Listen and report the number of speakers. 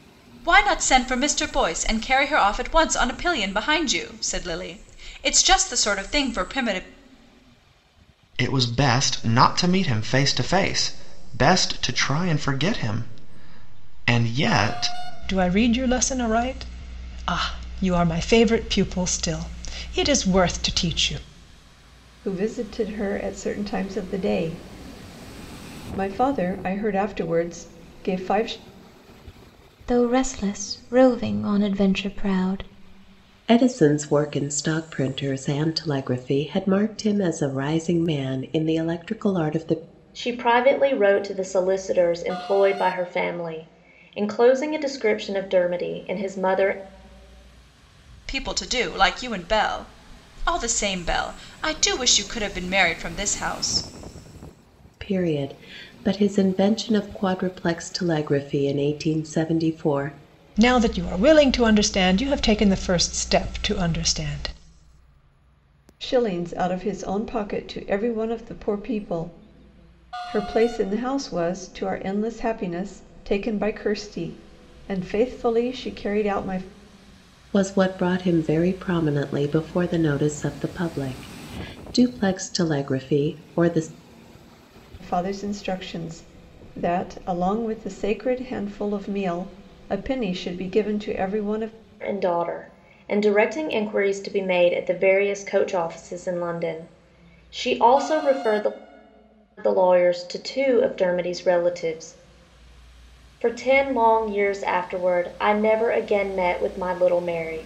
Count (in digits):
7